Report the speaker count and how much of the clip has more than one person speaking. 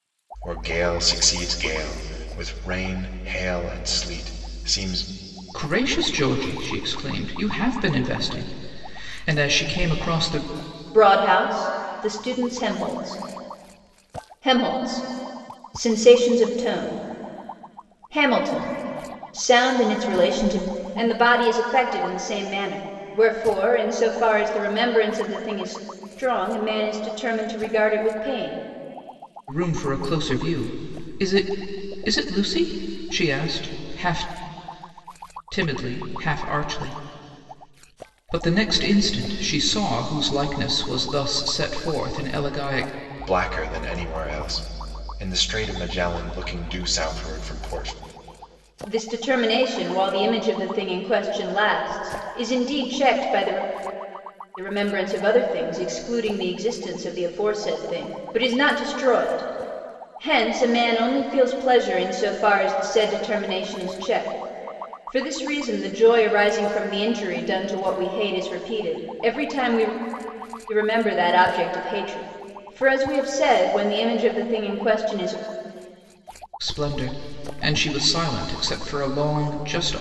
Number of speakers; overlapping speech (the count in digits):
3, no overlap